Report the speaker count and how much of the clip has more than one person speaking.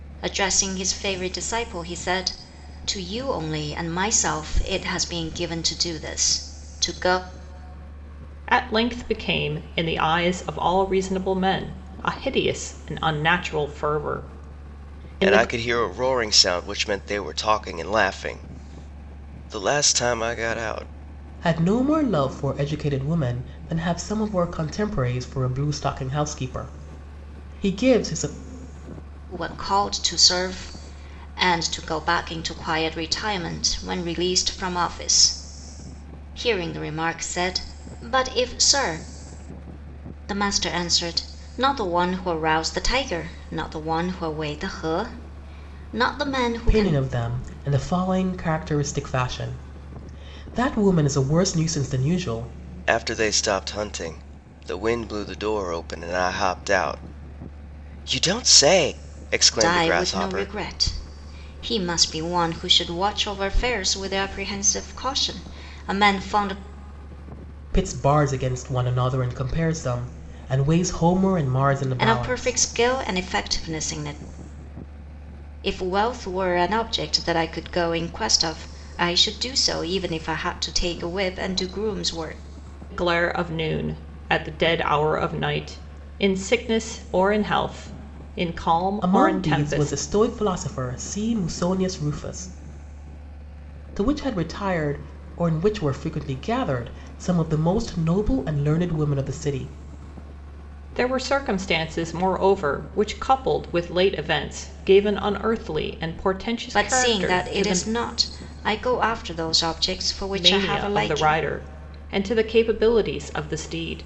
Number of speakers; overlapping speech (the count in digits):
4, about 5%